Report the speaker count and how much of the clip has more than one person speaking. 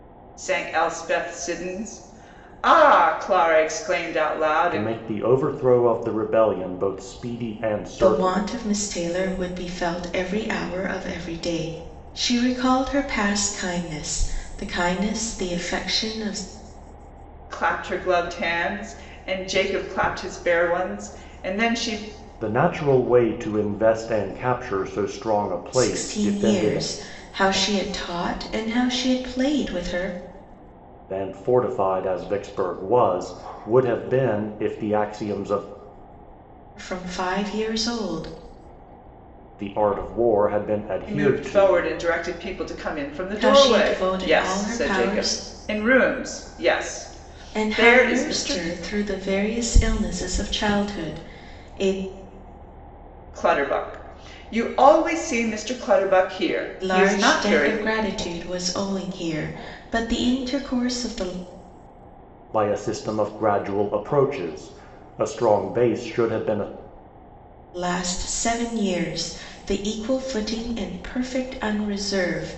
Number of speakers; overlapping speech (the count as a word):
three, about 9%